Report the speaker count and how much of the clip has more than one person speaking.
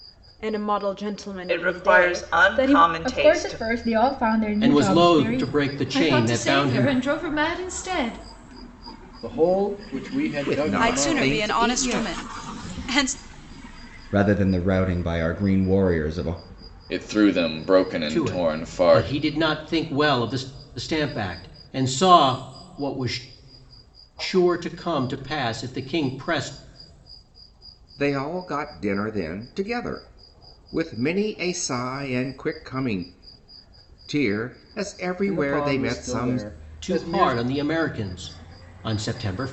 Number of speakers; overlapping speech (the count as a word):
ten, about 22%